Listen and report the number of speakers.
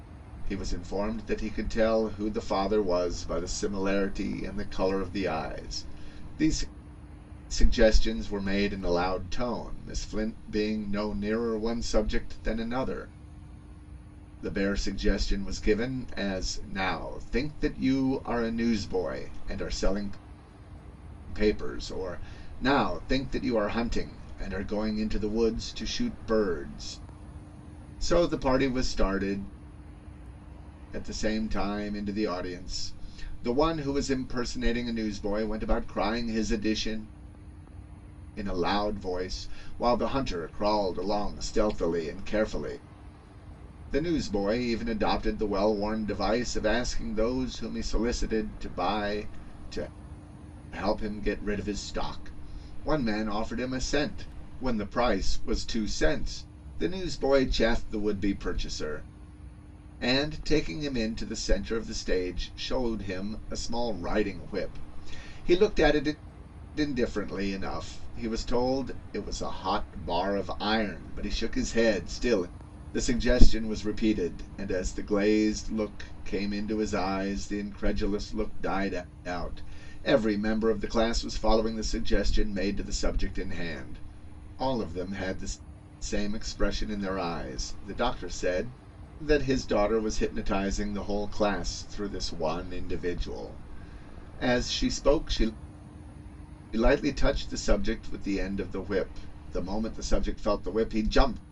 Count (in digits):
1